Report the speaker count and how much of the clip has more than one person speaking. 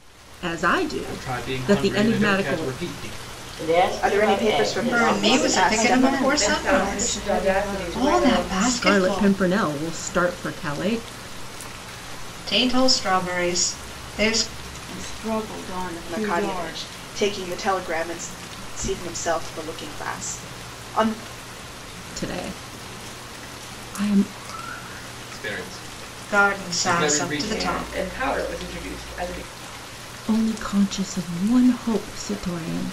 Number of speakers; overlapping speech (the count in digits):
7, about 29%